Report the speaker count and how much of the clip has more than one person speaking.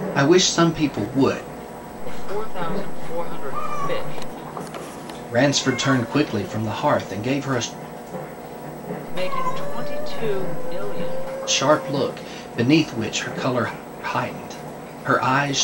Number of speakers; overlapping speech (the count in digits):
2, no overlap